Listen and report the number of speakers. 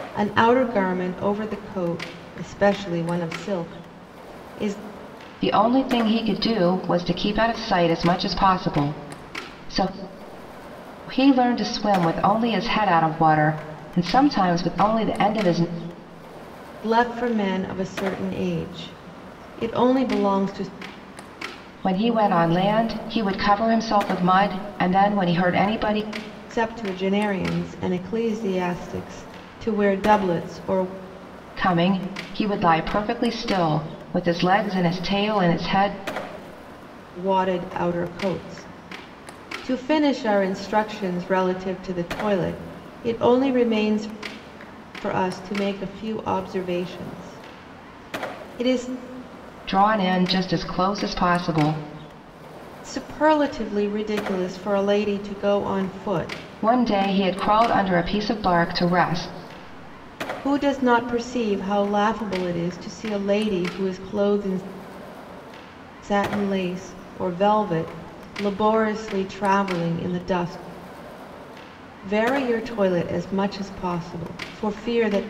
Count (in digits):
2